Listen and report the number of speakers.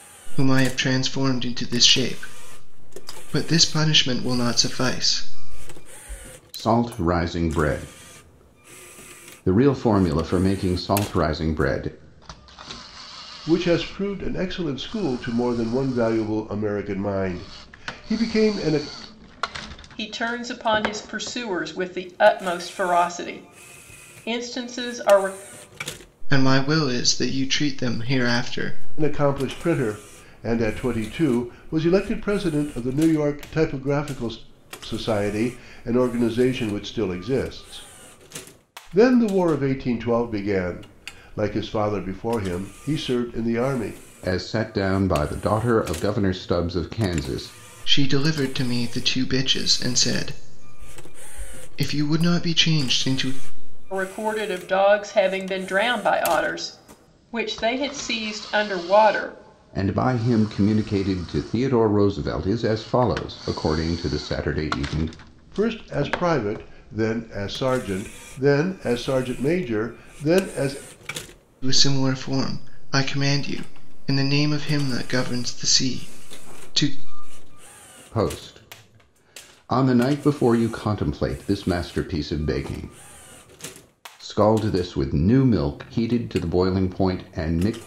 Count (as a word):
four